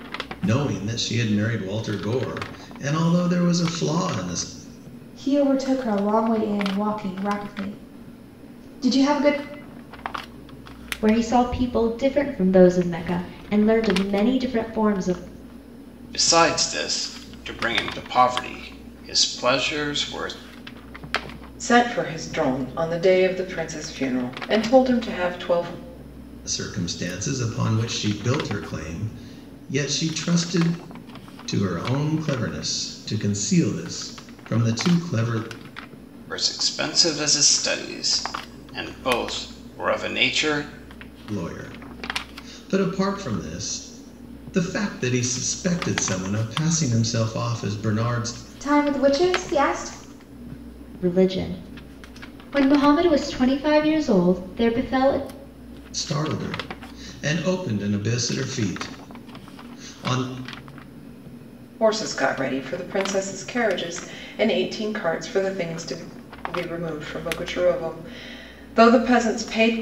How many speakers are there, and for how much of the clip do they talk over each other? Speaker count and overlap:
5, no overlap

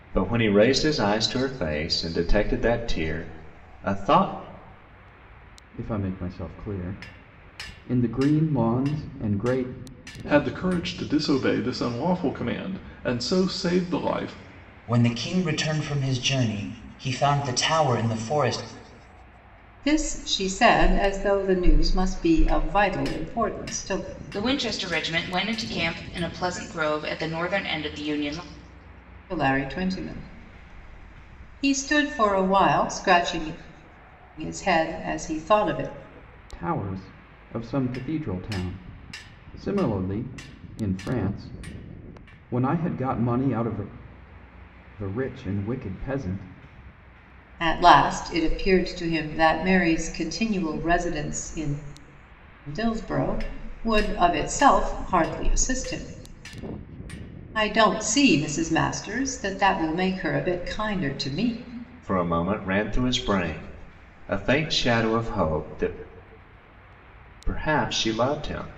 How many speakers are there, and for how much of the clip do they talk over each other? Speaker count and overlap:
6, no overlap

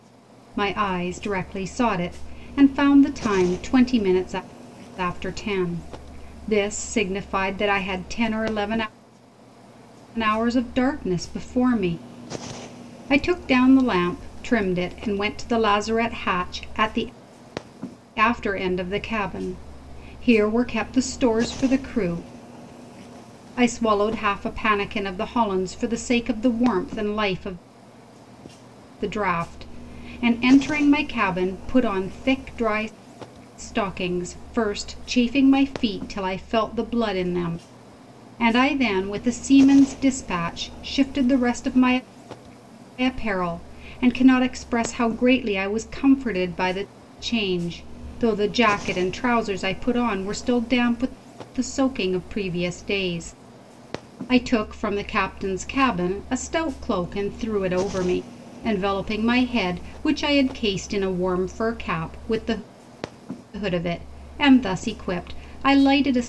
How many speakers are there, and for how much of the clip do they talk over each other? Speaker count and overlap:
1, no overlap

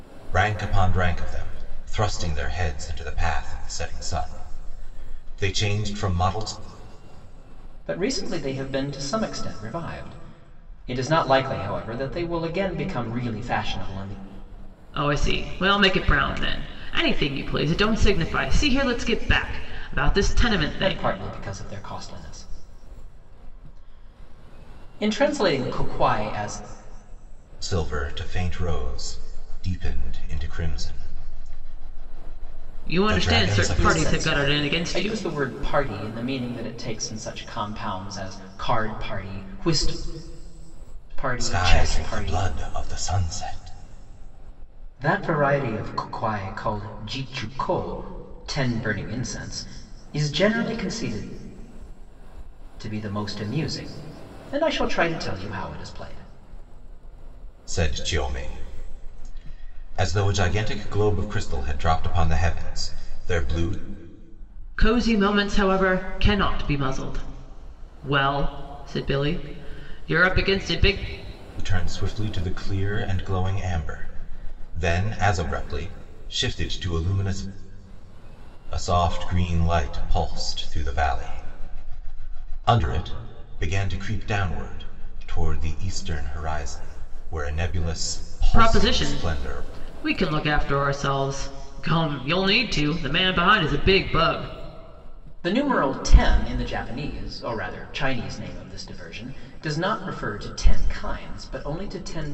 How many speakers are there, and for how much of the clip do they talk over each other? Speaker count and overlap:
3, about 5%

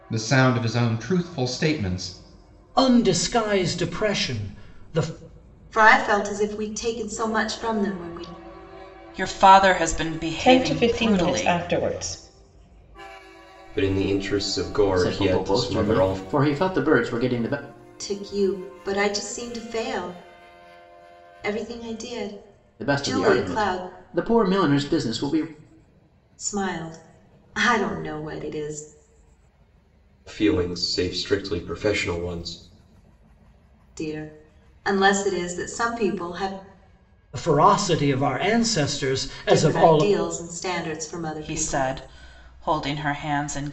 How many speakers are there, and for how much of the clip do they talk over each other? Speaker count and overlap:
7, about 11%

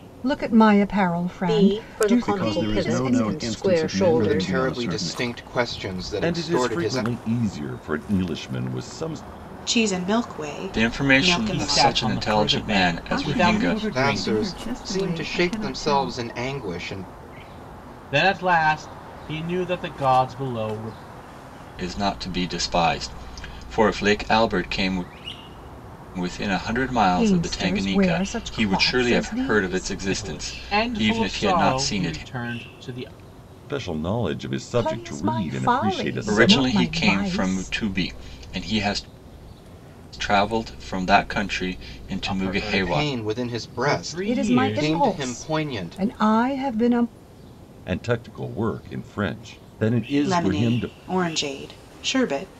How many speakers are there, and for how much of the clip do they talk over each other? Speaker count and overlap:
9, about 44%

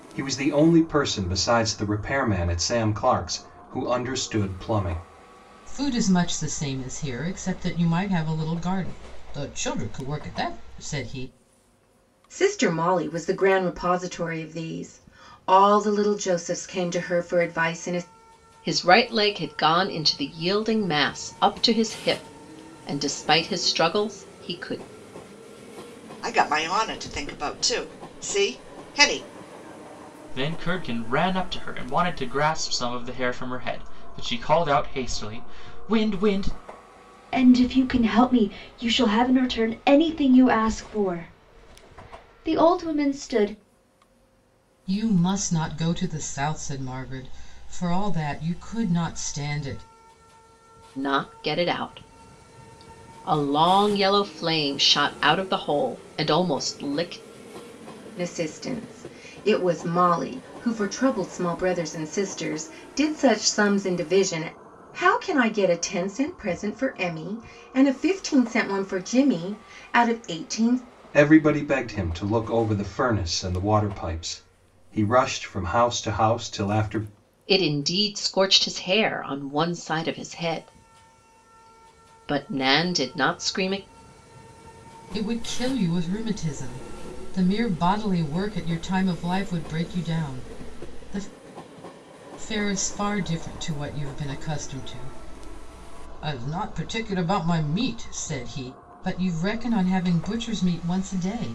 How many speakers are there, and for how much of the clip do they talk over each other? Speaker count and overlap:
7, no overlap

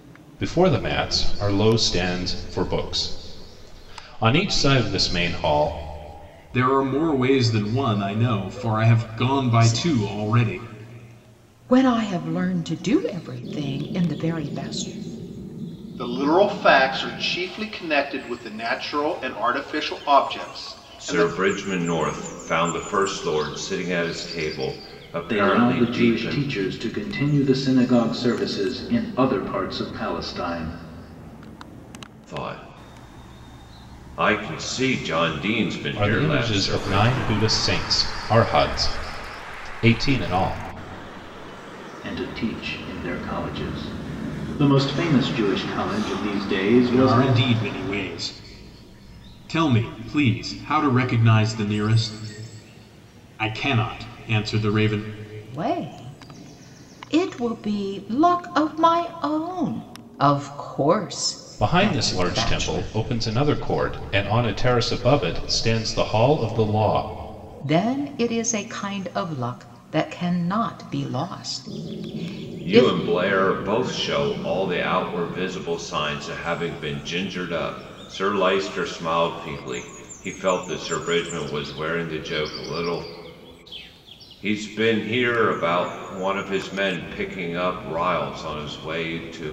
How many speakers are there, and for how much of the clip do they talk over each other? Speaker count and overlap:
6, about 7%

